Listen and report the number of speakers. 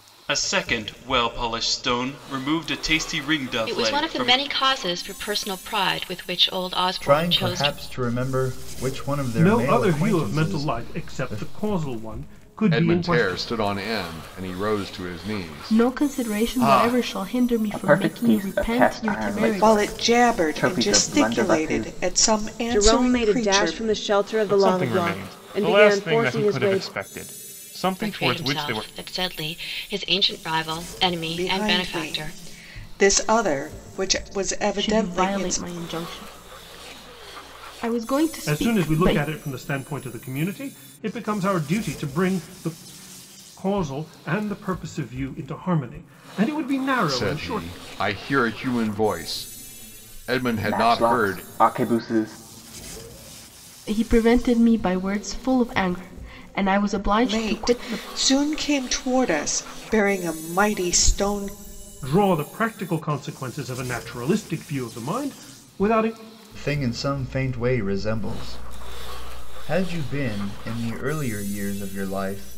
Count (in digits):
10